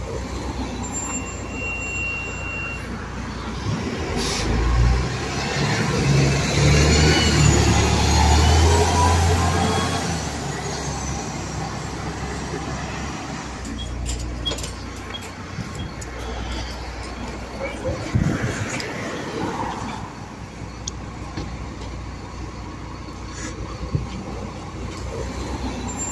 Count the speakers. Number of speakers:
zero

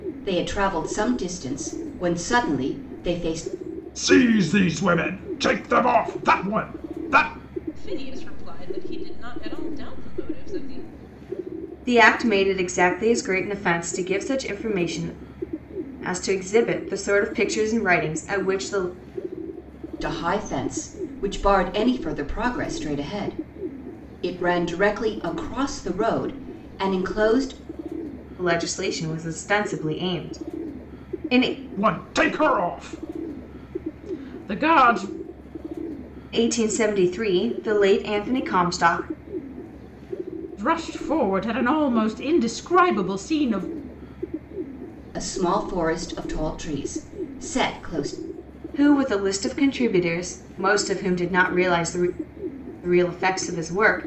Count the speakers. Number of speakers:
four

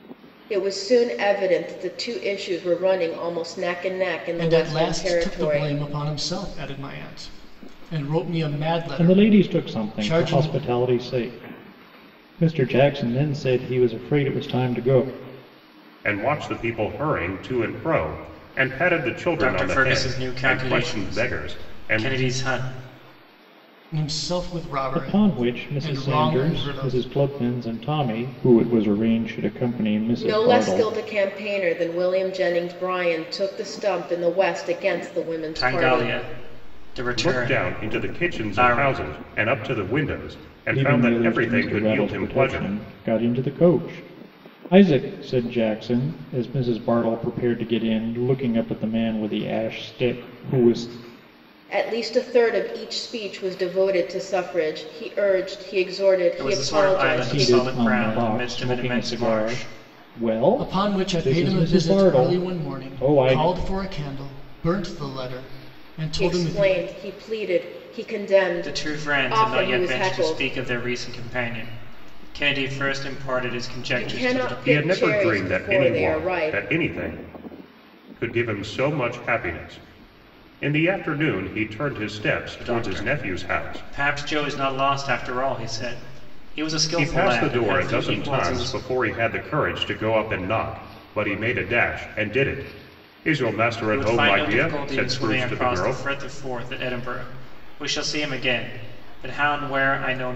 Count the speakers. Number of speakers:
five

